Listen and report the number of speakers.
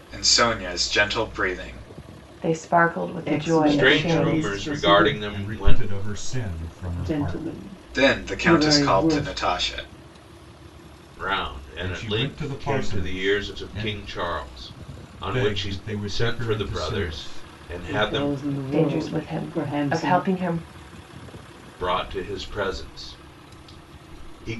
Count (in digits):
5